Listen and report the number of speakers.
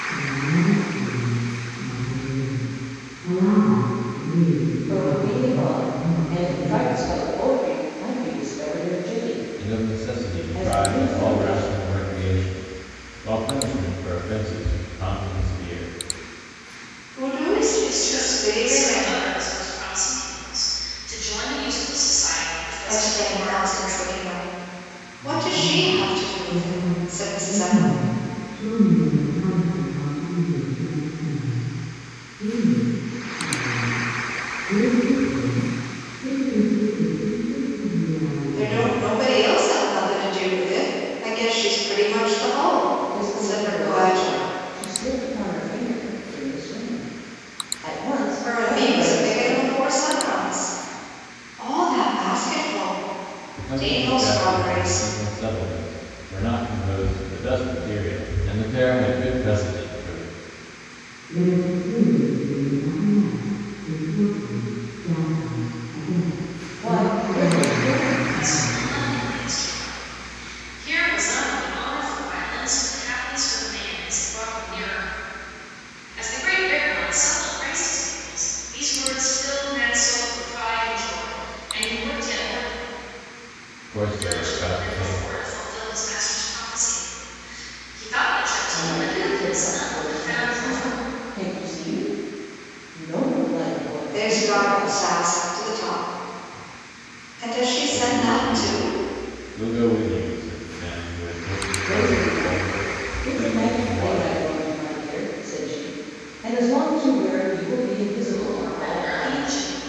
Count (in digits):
5